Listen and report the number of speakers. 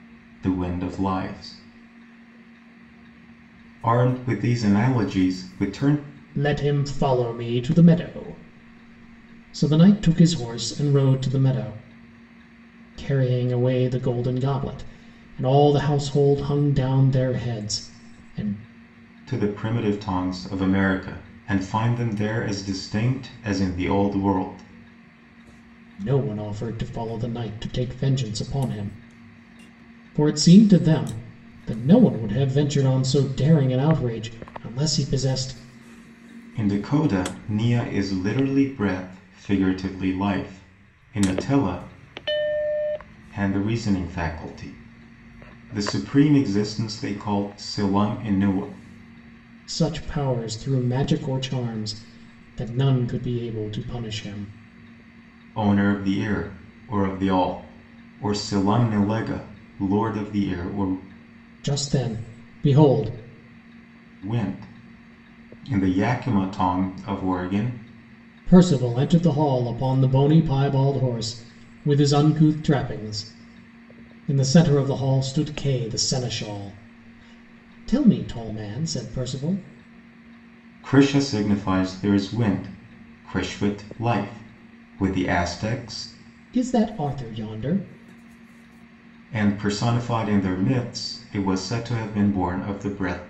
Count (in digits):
2